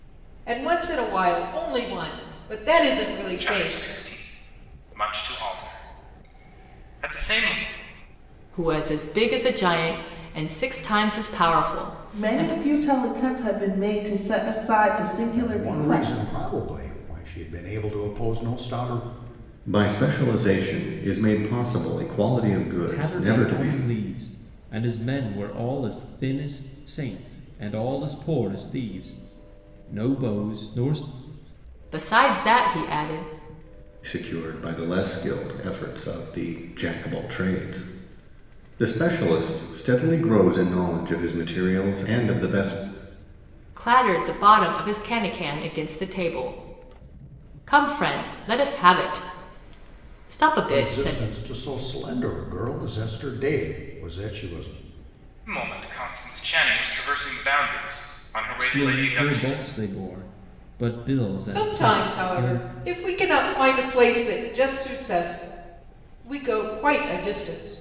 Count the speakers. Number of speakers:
7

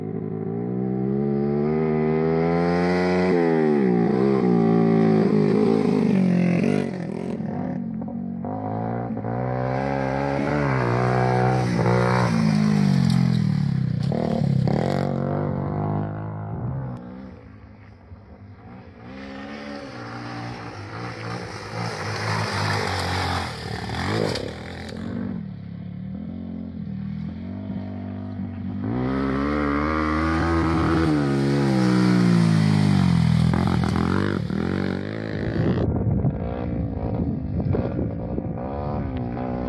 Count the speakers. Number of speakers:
0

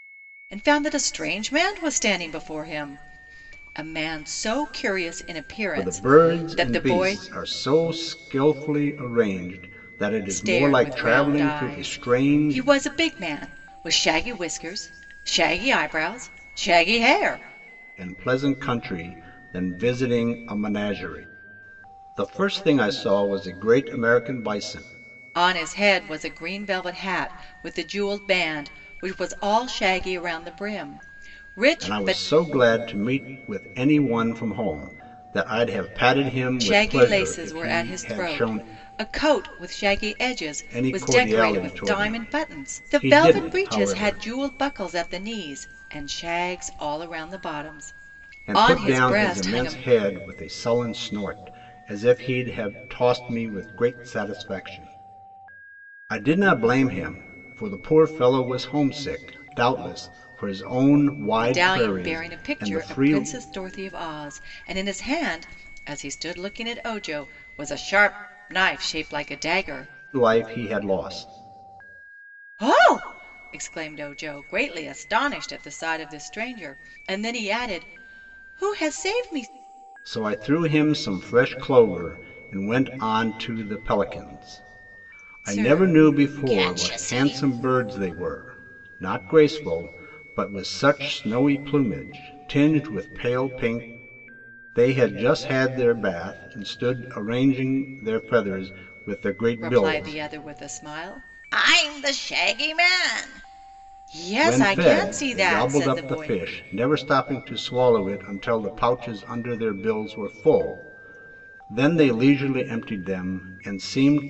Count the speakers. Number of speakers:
2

